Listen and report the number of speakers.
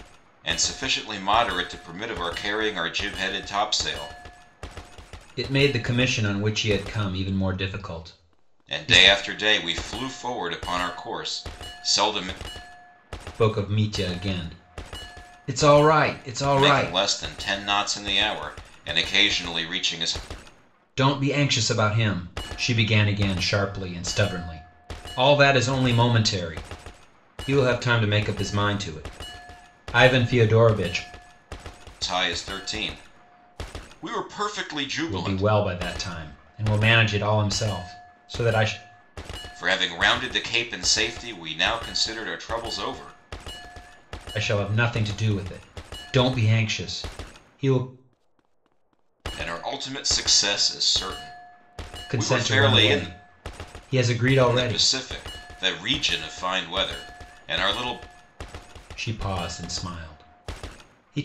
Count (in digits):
2